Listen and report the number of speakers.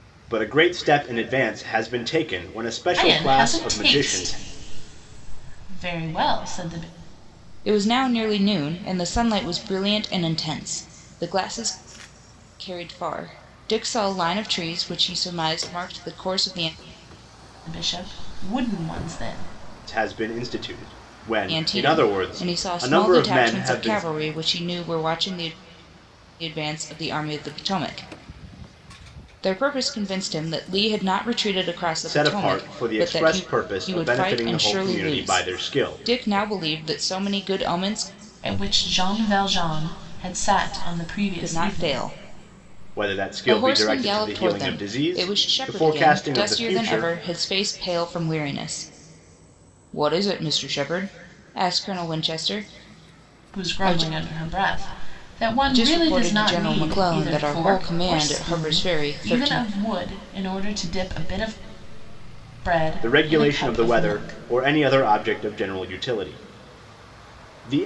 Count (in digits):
3